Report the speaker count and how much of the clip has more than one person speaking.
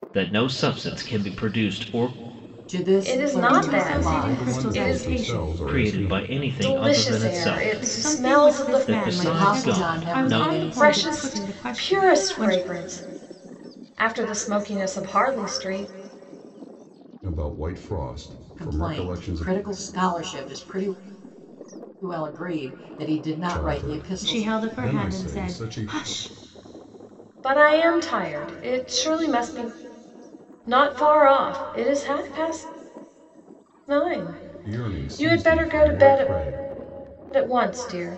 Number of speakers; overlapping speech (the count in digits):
5, about 37%